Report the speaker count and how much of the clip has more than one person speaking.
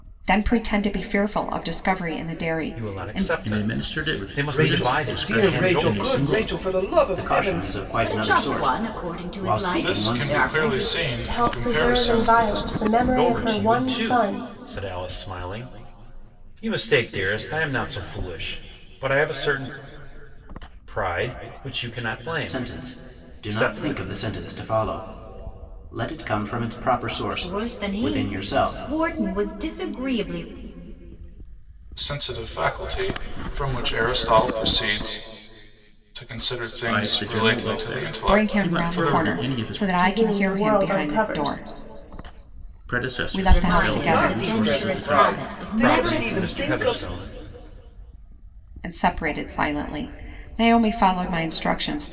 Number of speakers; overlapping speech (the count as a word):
eight, about 42%